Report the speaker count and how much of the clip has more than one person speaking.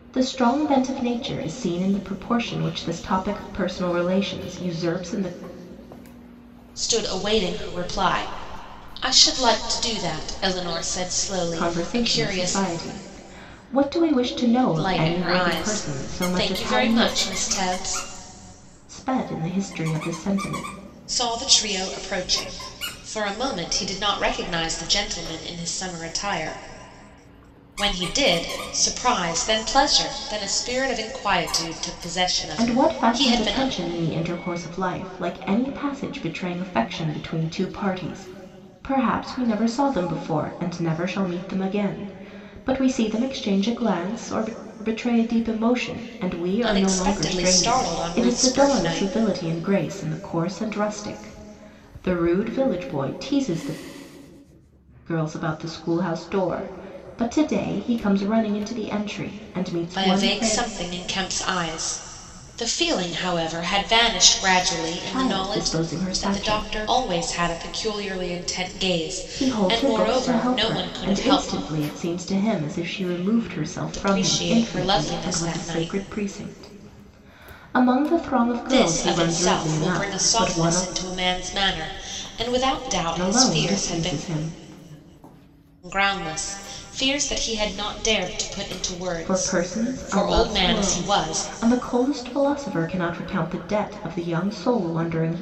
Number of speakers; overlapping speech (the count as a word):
two, about 20%